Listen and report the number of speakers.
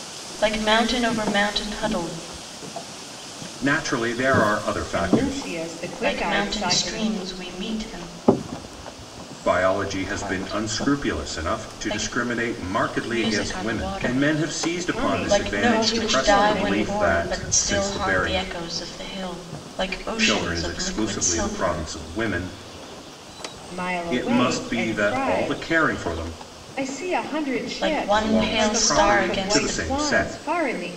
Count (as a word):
three